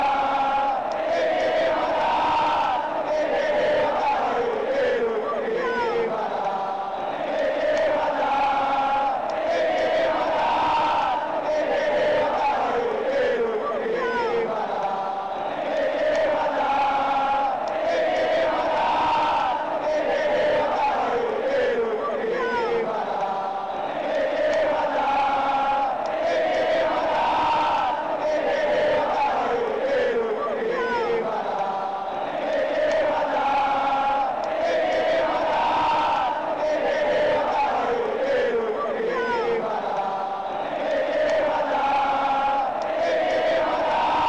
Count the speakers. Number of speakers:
0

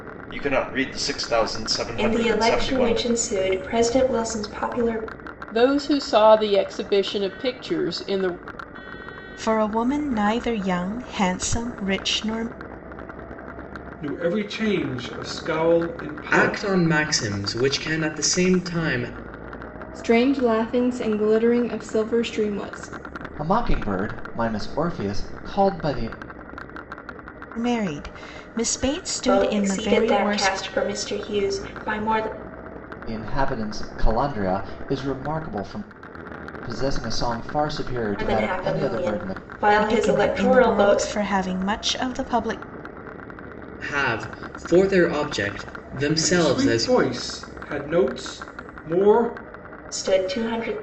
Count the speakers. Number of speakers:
8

